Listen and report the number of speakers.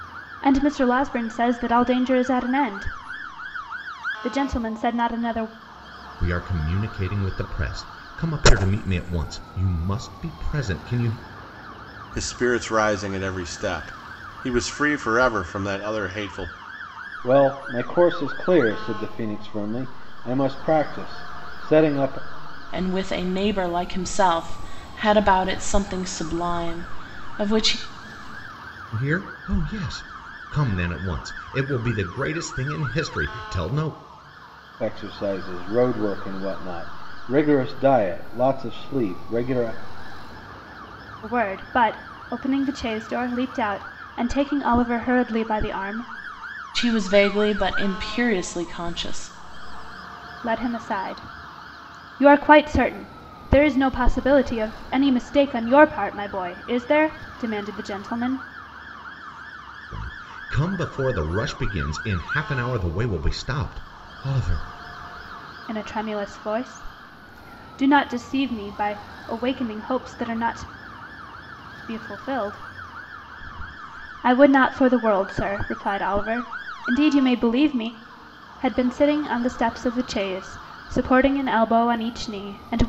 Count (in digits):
5